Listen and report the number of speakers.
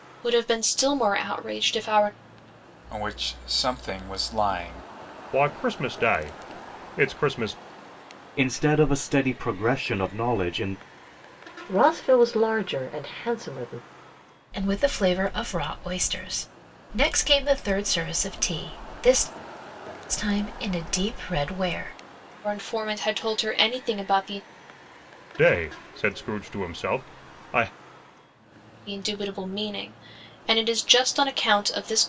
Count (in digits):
6